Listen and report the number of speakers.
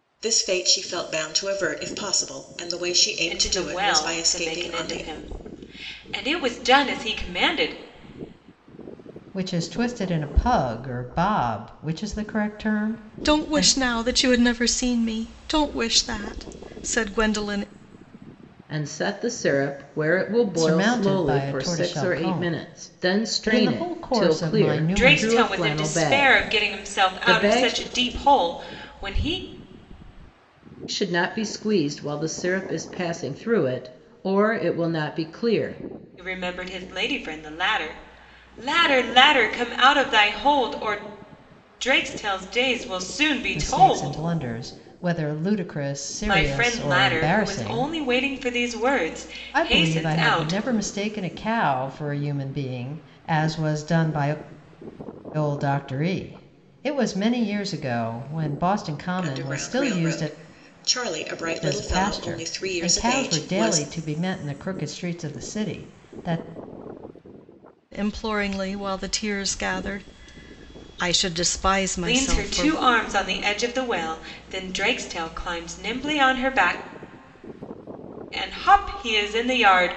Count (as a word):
five